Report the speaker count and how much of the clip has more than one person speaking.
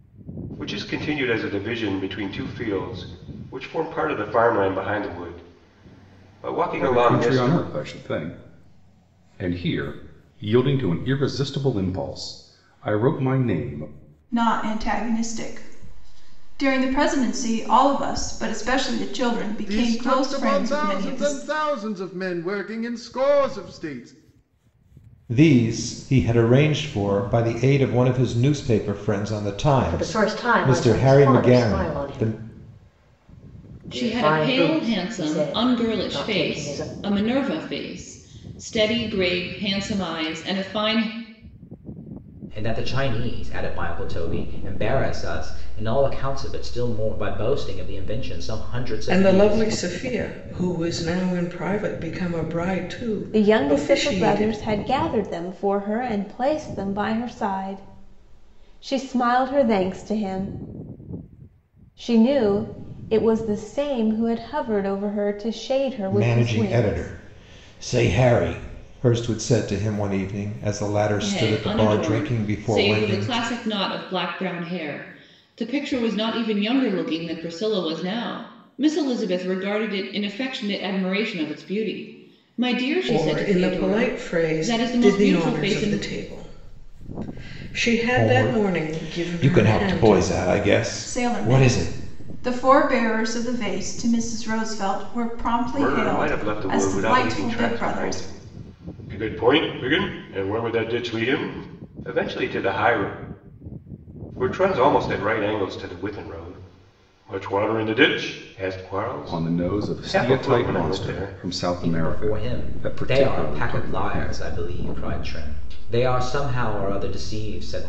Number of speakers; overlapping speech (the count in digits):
10, about 23%